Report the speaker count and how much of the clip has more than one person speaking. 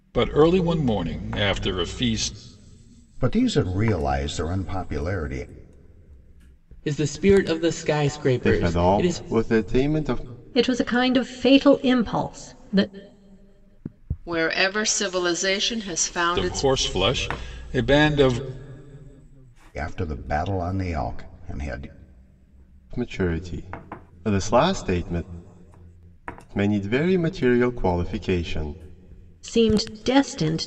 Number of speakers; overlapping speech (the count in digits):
6, about 4%